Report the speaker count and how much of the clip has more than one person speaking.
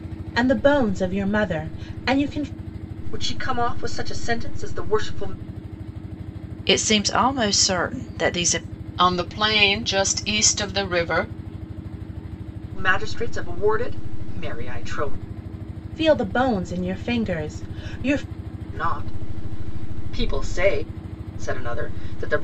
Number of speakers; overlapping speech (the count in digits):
4, no overlap